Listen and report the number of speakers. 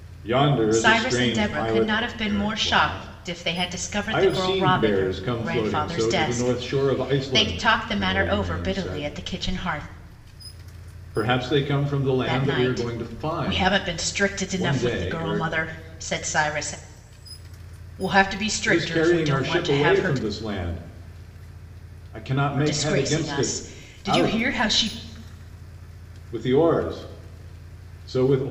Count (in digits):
2